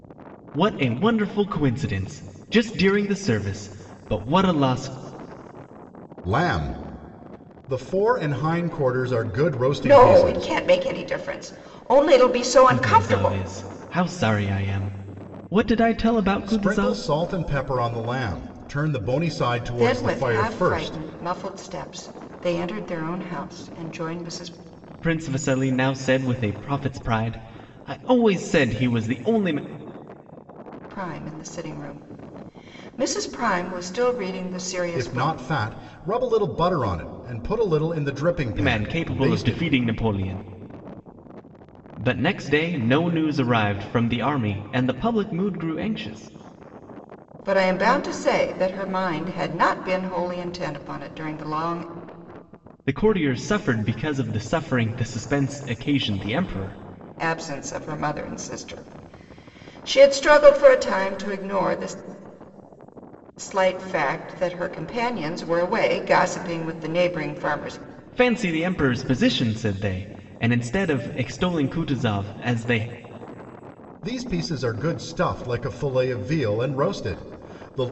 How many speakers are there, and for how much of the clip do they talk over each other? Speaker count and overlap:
three, about 7%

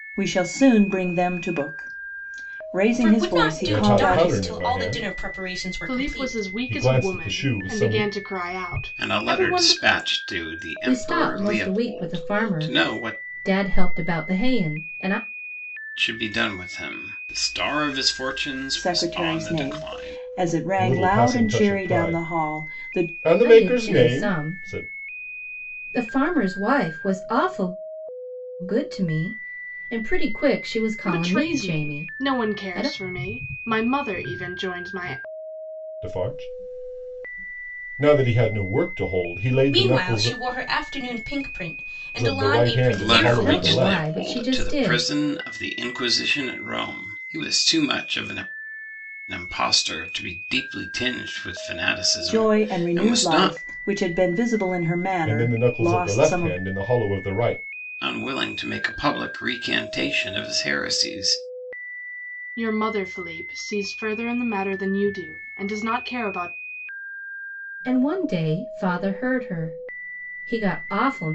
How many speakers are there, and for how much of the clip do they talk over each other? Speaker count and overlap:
six, about 31%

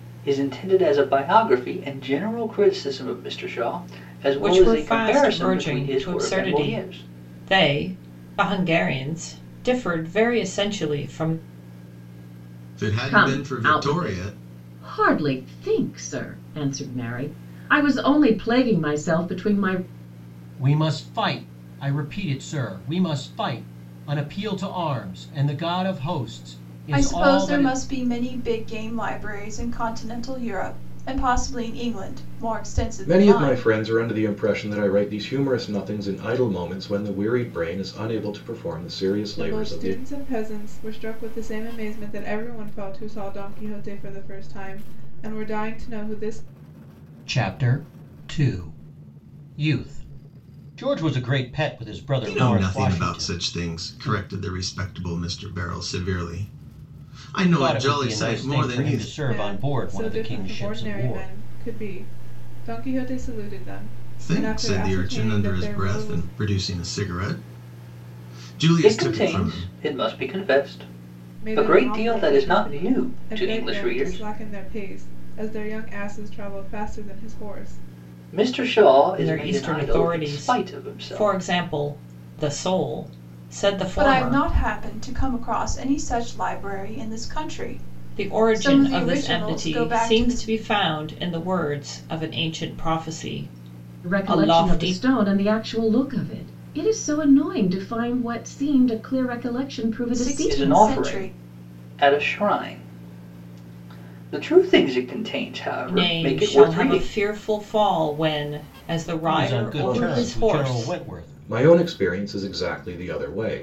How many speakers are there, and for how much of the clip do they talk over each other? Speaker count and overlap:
eight, about 25%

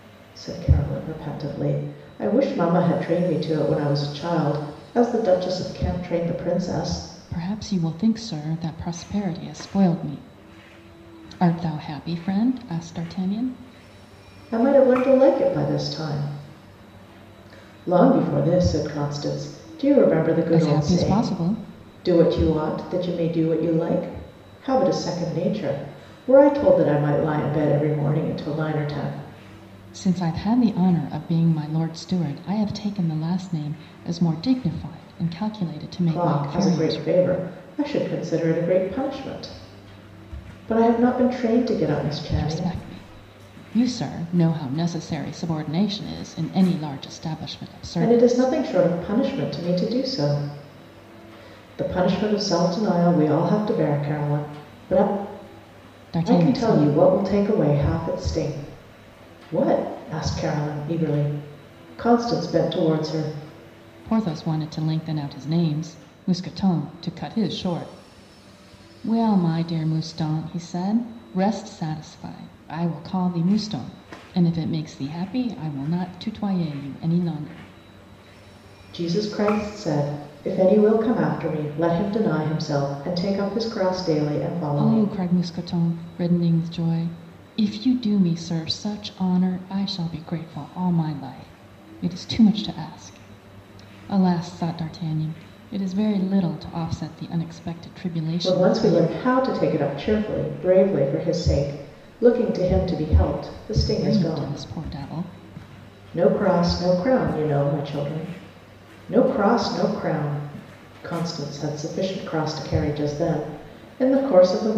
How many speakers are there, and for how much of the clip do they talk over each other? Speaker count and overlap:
two, about 5%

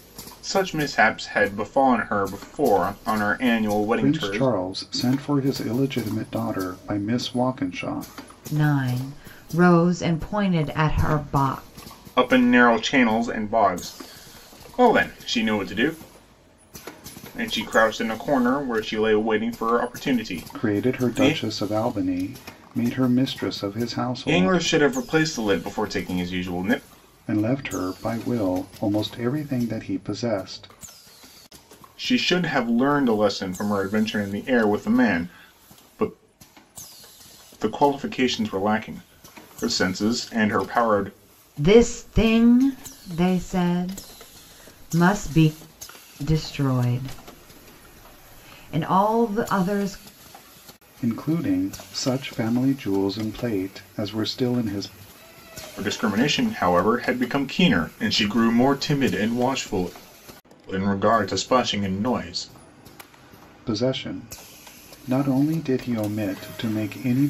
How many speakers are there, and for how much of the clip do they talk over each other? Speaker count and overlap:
three, about 3%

